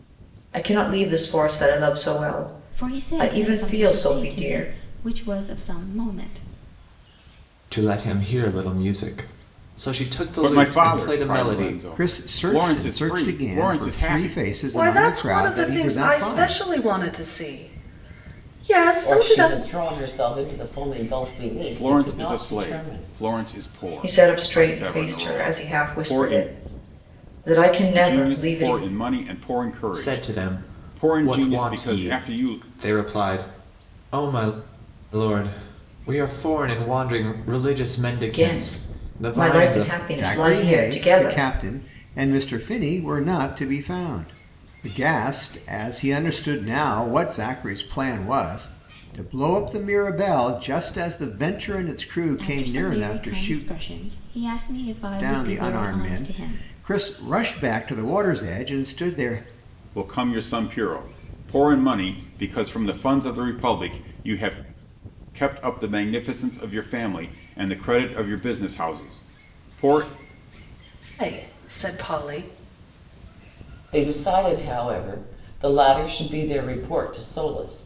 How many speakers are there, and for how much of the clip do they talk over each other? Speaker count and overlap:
seven, about 28%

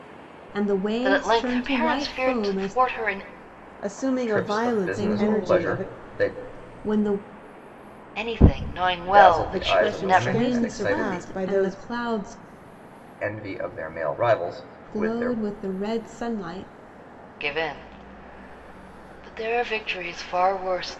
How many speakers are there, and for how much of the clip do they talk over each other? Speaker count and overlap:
four, about 35%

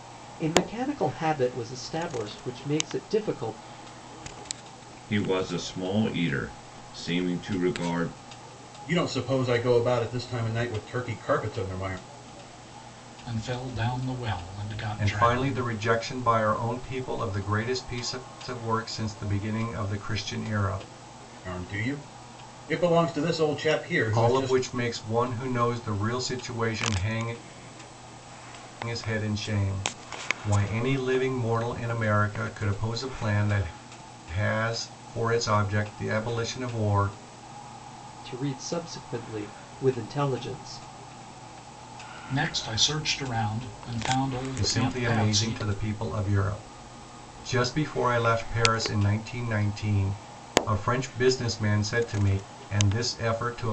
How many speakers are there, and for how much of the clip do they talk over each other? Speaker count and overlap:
five, about 4%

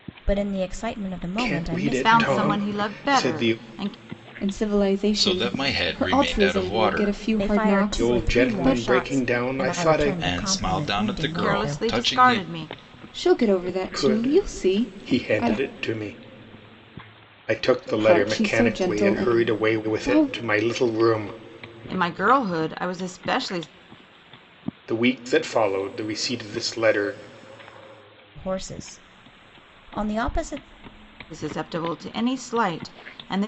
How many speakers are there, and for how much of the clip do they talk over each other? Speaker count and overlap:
five, about 40%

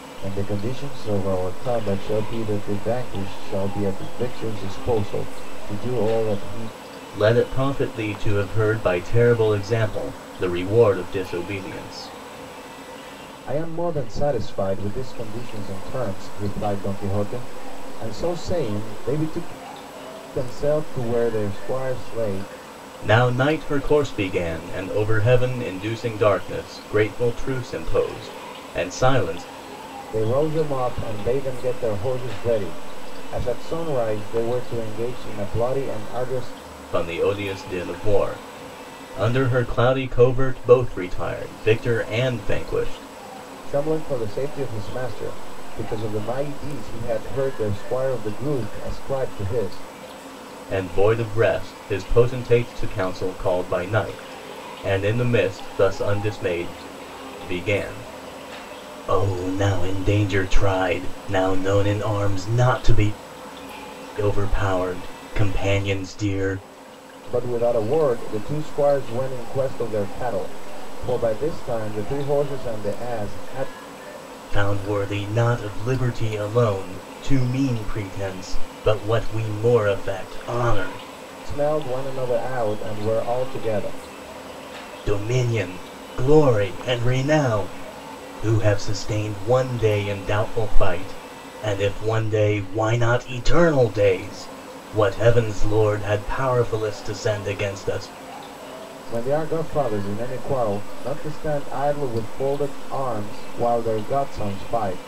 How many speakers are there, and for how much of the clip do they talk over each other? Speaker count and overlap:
two, no overlap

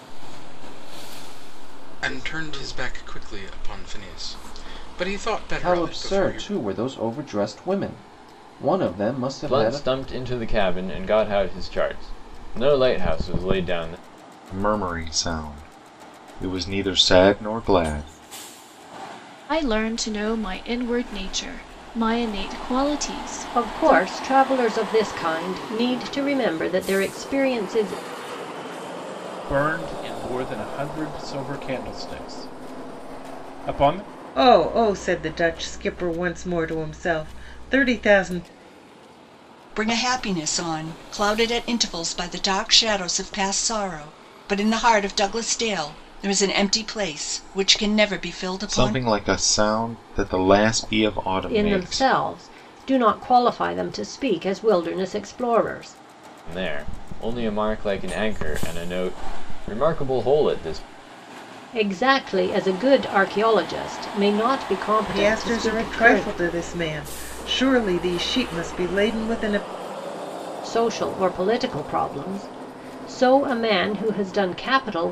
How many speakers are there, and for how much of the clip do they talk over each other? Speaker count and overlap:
ten, about 7%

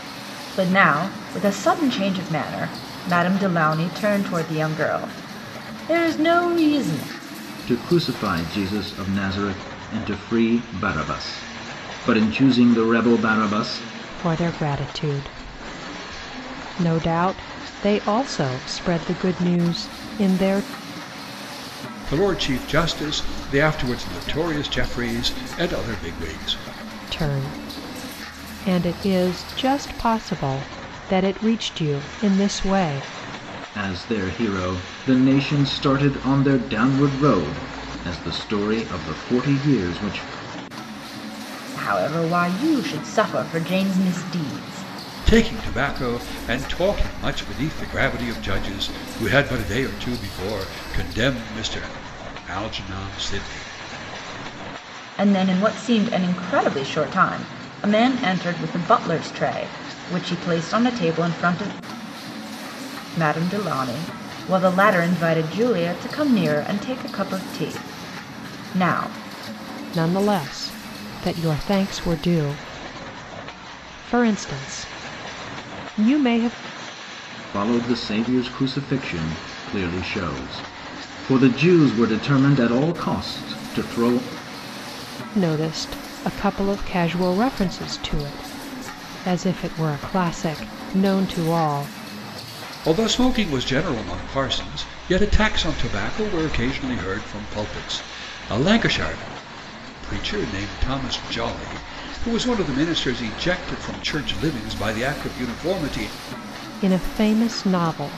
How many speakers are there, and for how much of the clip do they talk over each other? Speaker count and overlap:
four, no overlap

